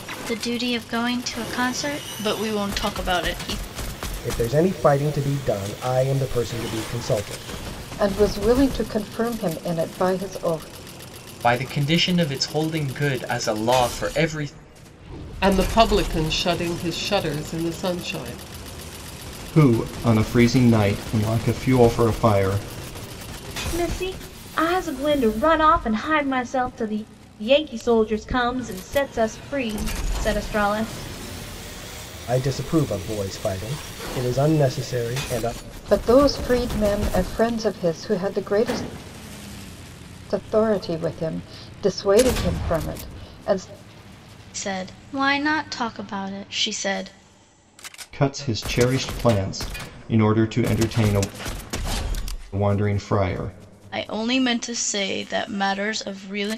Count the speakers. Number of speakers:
7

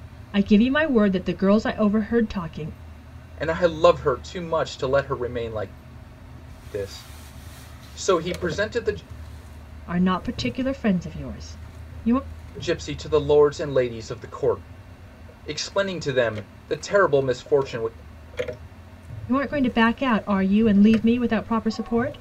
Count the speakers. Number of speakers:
2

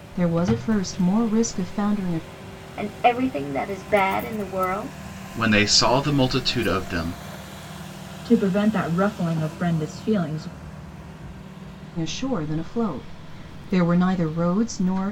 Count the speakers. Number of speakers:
4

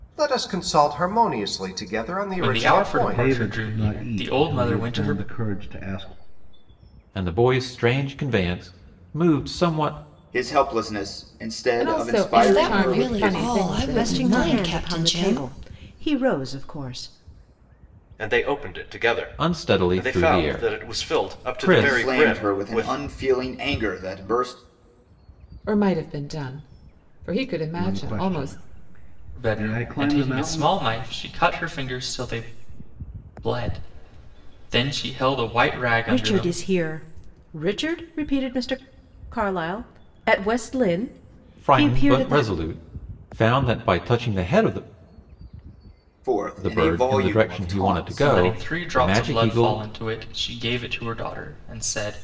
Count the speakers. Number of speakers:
9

